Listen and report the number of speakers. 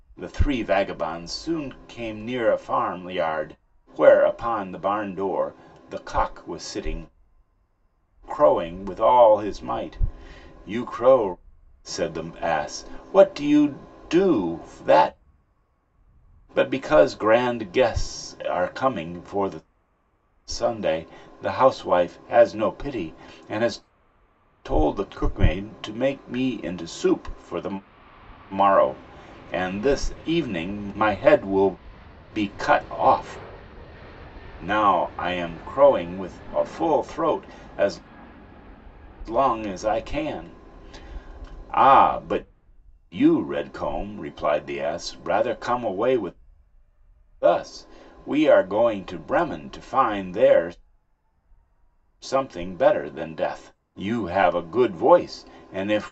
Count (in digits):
1